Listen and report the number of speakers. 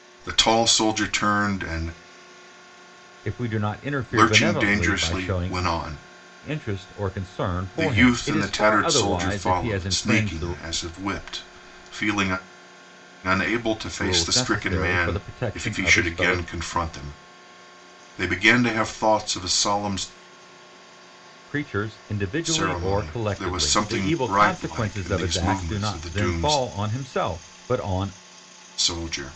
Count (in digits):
2